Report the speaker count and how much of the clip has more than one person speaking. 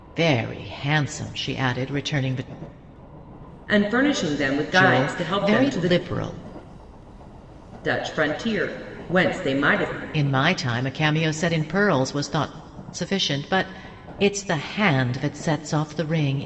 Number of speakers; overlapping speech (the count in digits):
2, about 8%